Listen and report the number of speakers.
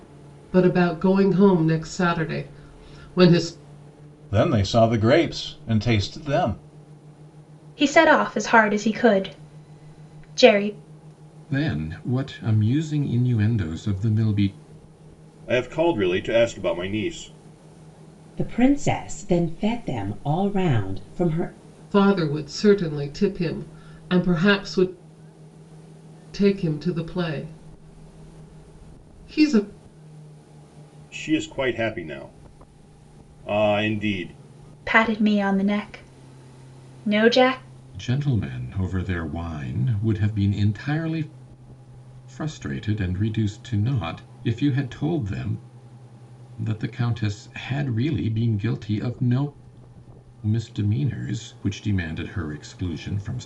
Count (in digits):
6